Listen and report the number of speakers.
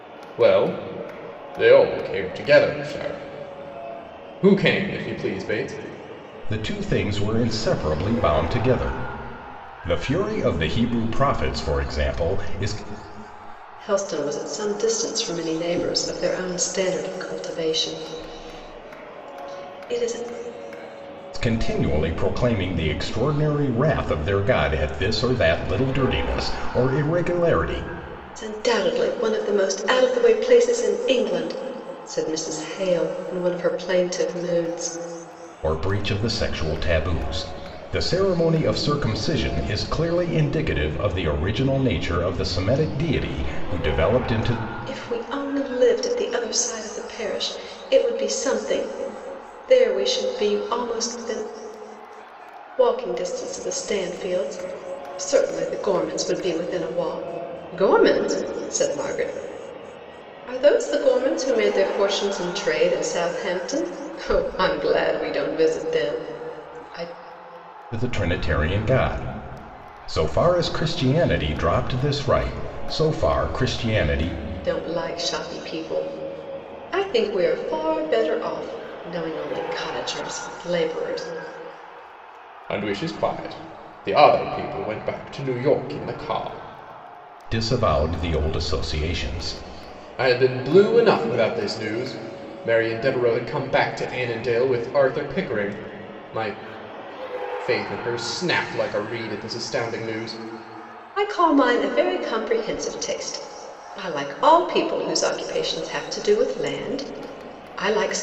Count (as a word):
three